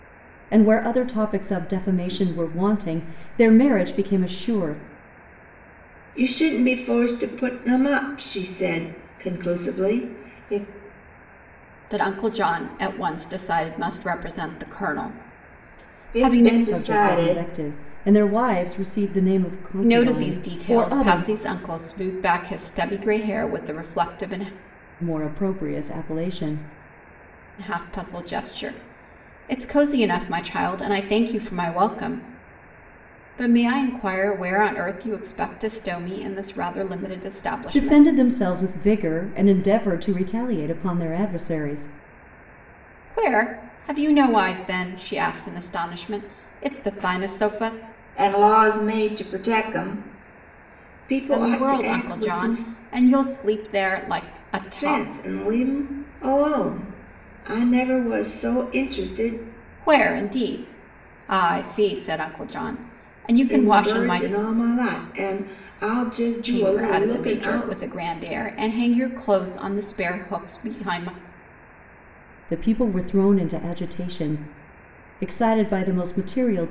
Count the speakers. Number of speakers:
three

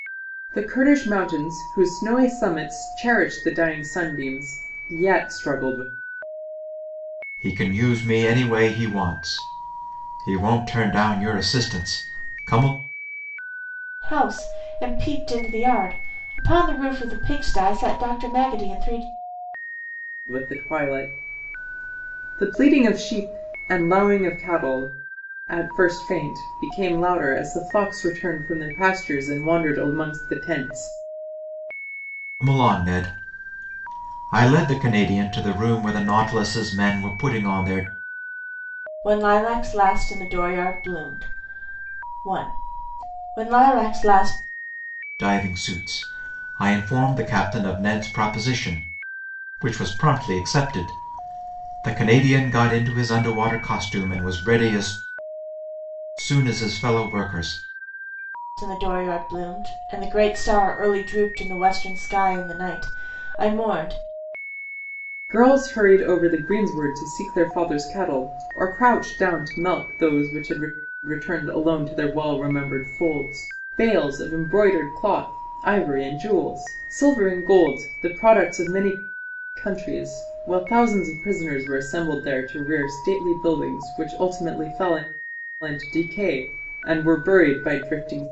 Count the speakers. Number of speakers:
three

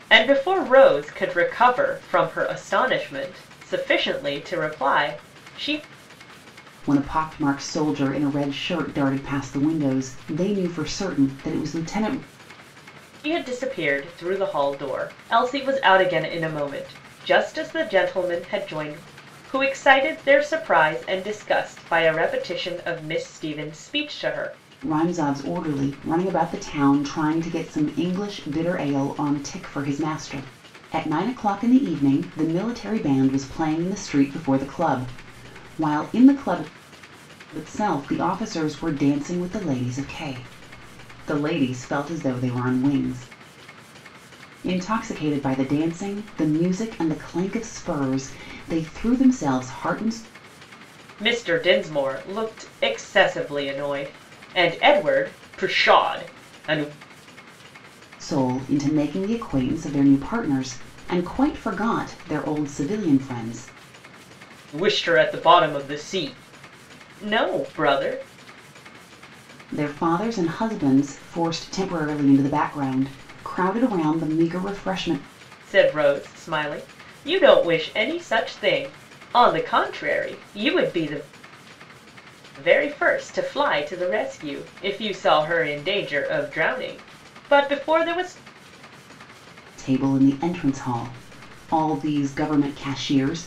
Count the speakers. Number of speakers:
two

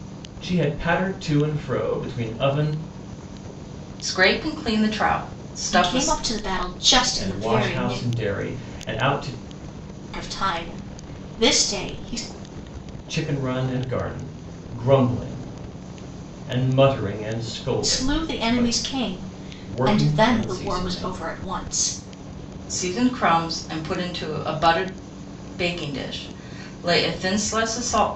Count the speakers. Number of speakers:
three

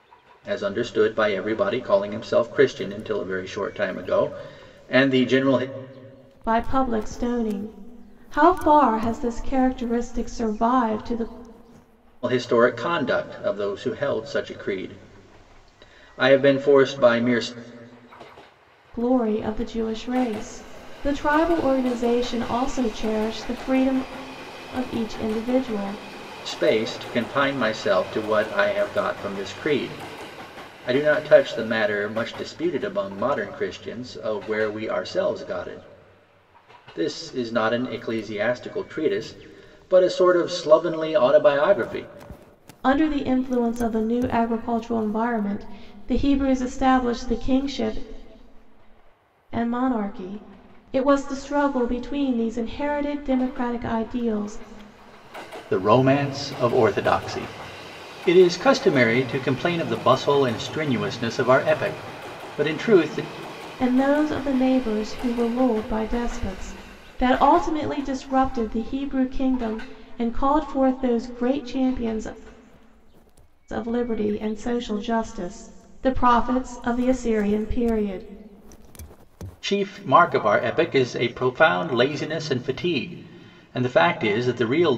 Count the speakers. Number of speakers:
two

